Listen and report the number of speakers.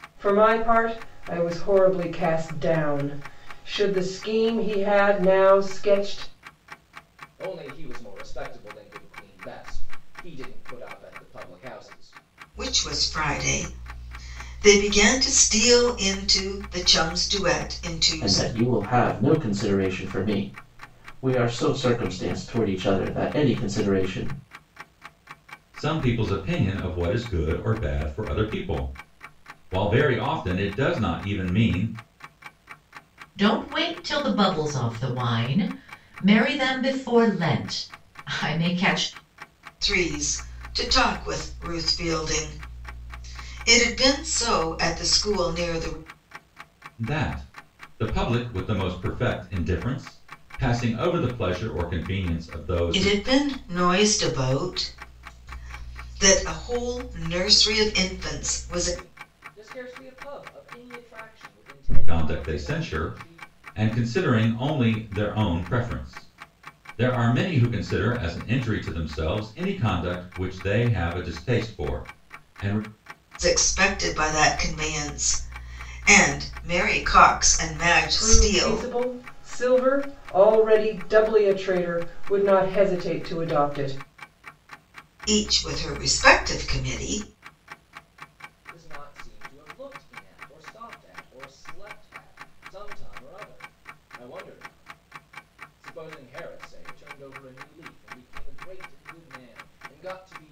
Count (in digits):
6